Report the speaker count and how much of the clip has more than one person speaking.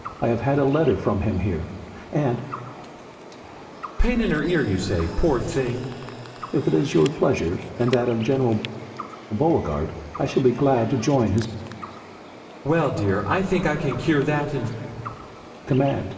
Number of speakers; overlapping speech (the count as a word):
two, no overlap